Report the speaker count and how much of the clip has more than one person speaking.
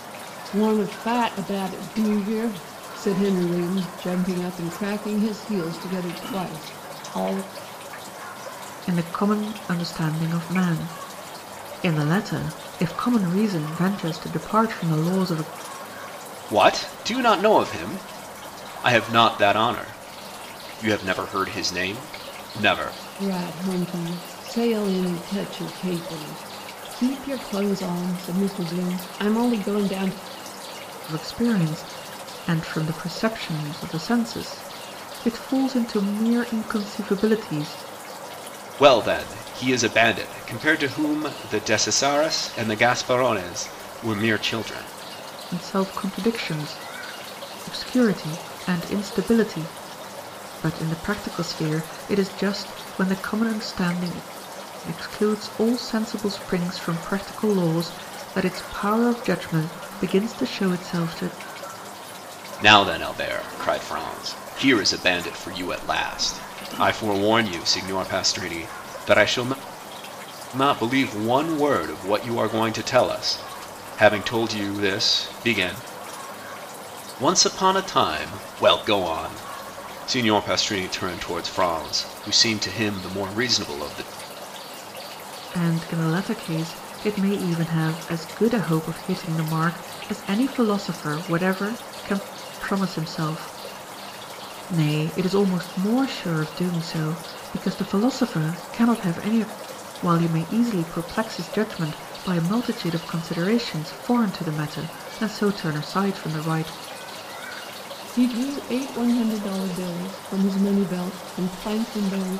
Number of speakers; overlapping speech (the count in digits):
3, no overlap